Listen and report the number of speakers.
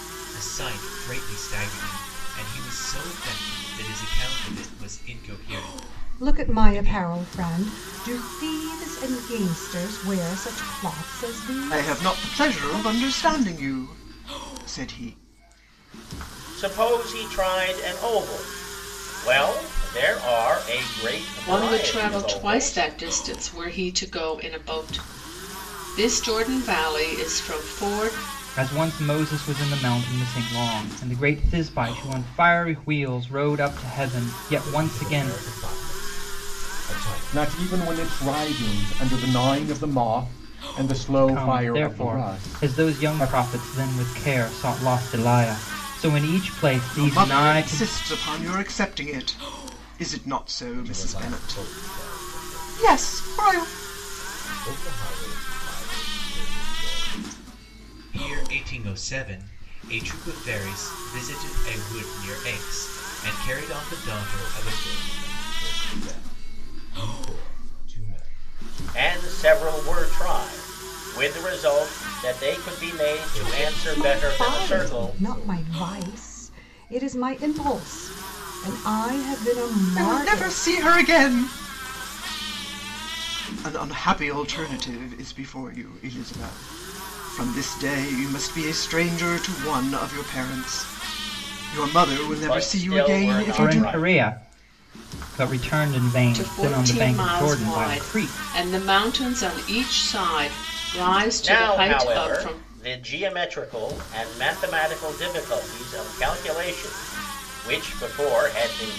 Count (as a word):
eight